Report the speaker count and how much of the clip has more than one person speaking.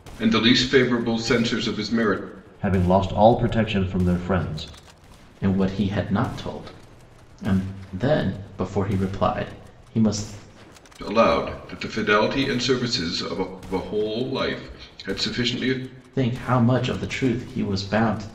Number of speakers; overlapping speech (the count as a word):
three, no overlap